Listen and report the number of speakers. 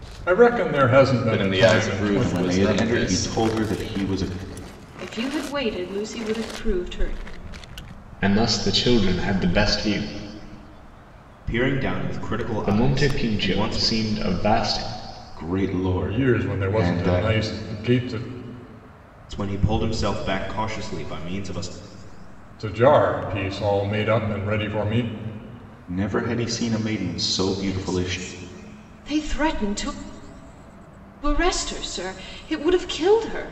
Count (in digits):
6